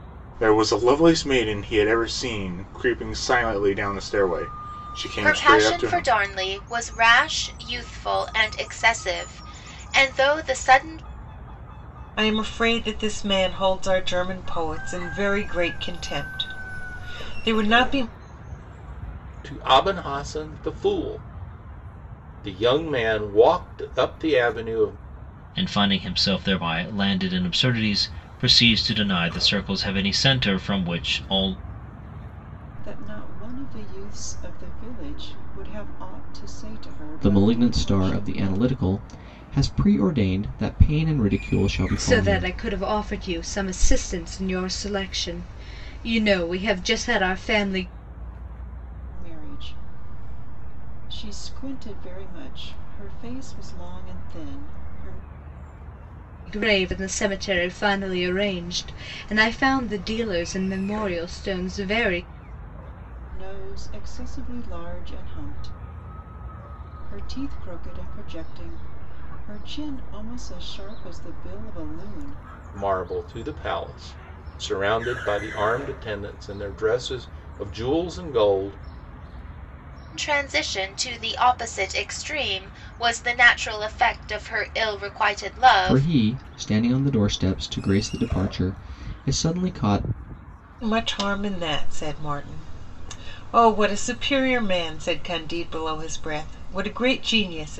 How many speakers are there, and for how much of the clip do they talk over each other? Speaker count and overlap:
8, about 3%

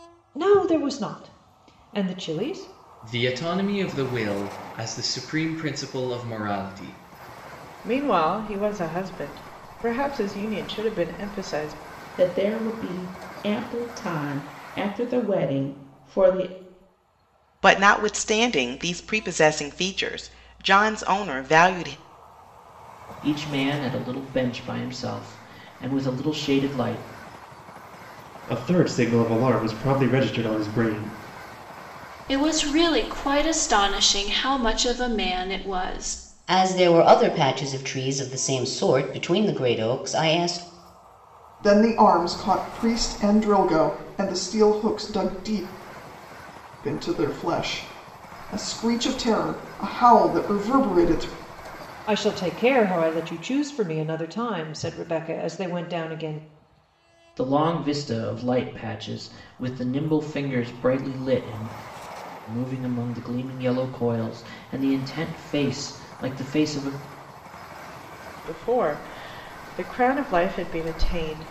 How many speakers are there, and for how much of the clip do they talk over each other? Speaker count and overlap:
10, no overlap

